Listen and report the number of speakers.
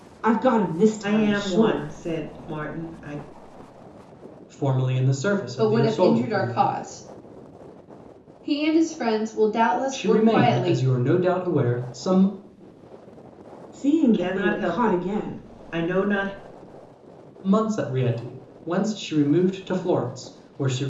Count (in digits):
4